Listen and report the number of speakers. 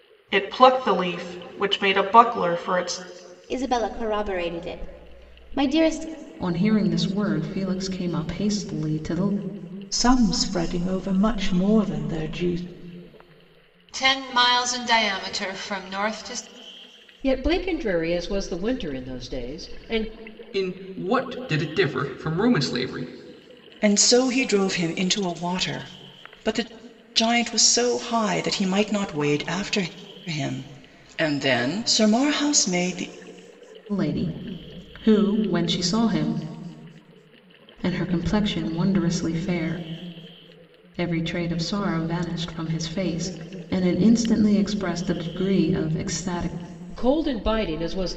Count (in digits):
8